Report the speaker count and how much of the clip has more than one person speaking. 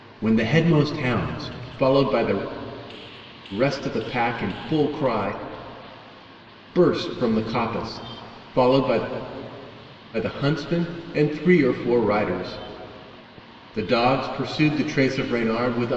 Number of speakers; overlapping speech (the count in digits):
1, no overlap